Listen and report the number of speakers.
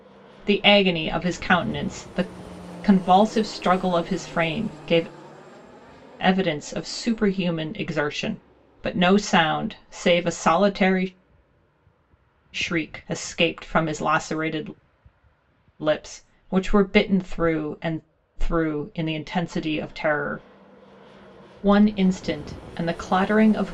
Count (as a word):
one